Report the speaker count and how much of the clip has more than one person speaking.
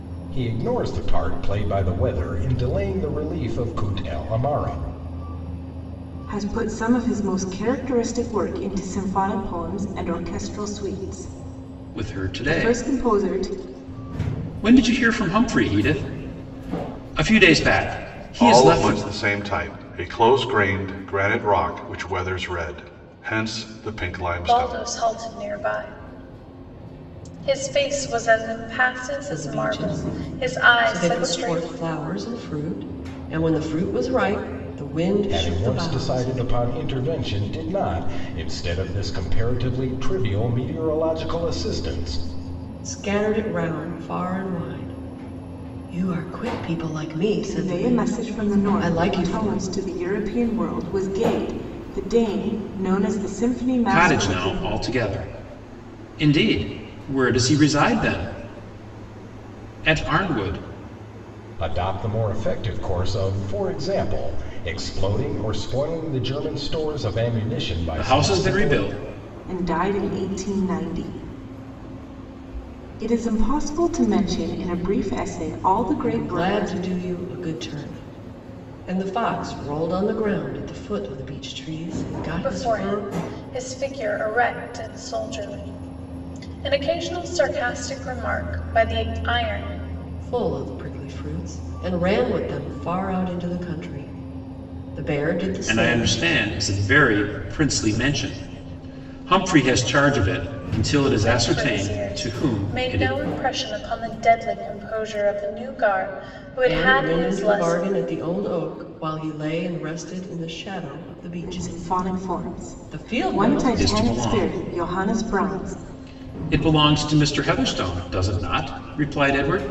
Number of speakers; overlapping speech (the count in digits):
6, about 17%